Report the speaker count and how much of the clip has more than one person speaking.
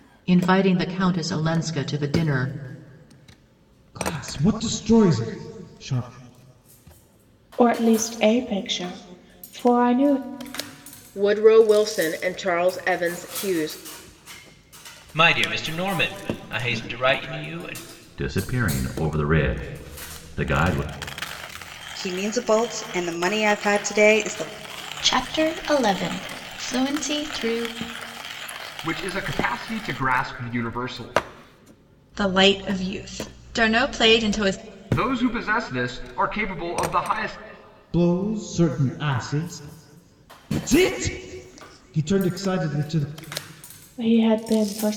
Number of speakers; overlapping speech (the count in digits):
10, no overlap